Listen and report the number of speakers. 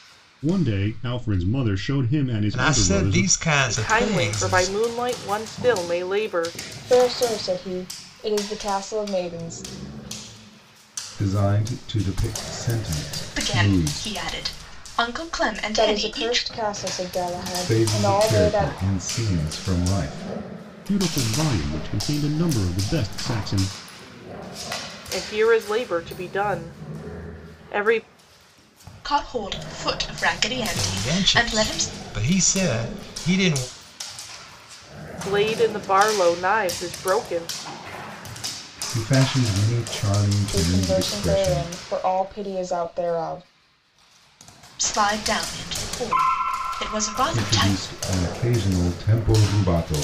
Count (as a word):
six